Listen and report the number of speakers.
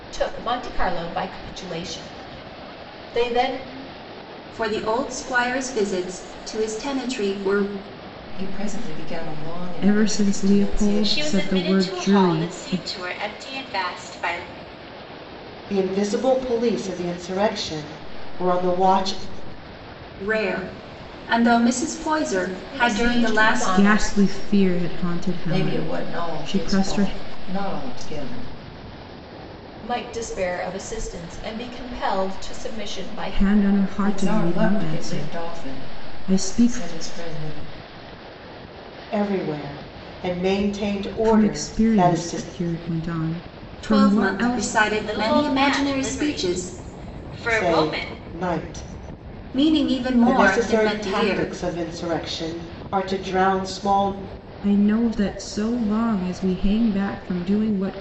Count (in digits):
7